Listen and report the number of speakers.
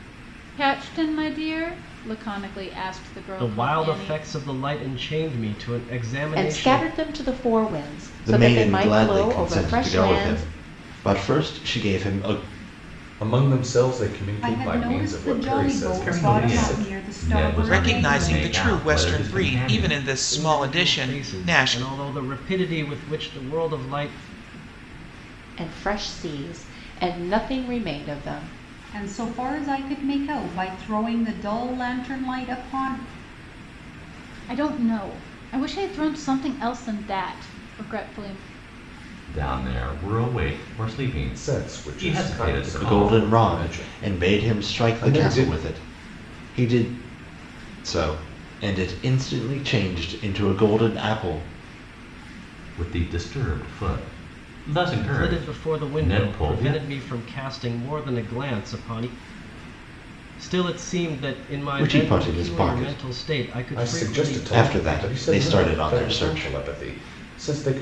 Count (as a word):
eight